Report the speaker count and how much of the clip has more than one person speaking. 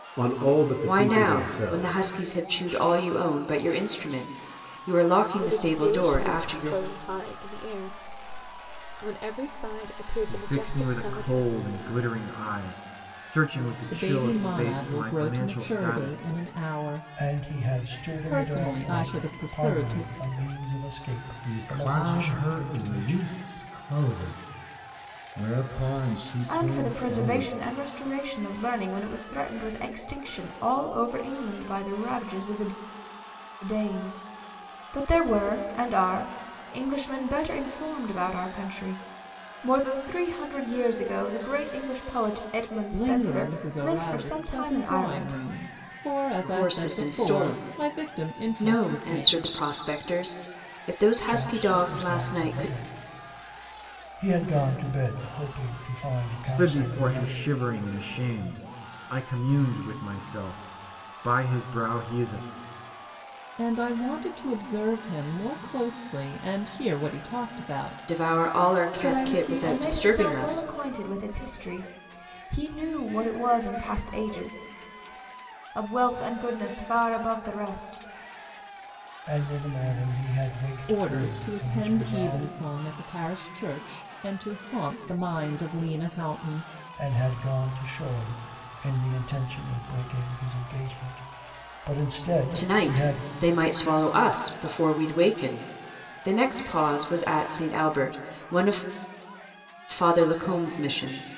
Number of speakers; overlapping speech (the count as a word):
eight, about 25%